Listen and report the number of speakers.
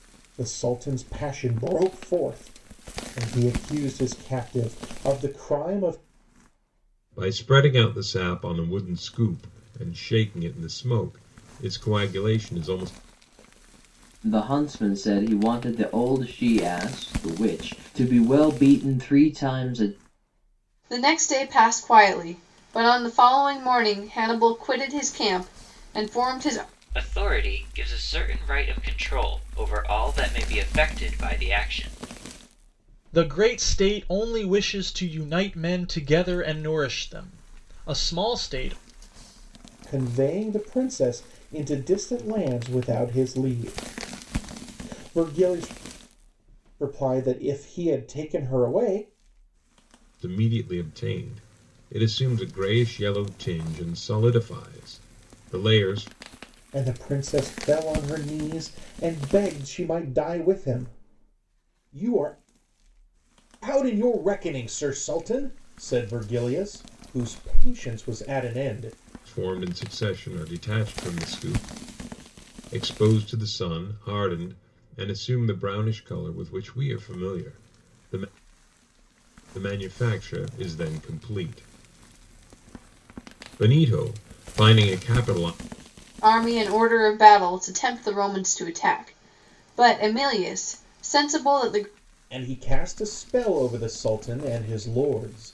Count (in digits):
6